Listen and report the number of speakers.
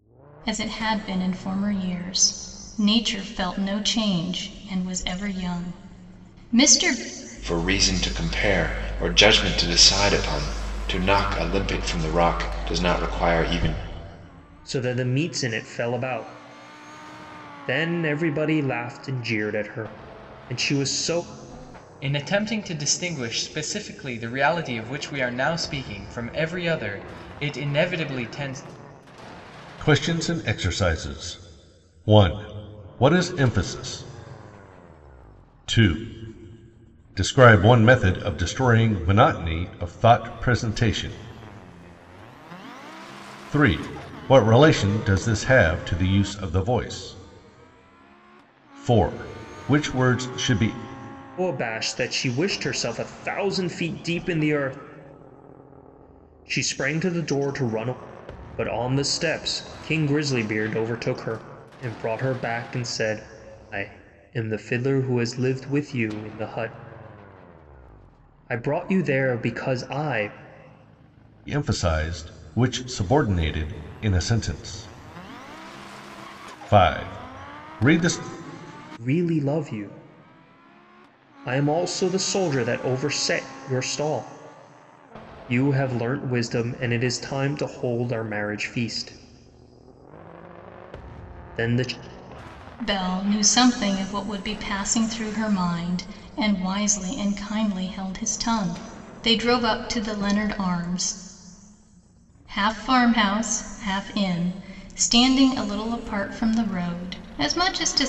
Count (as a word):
five